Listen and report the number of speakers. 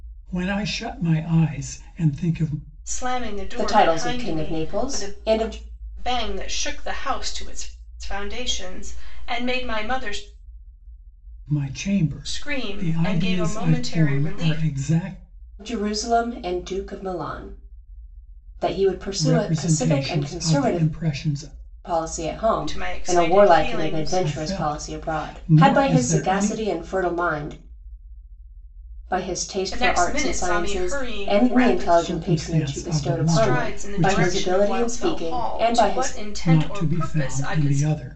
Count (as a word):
three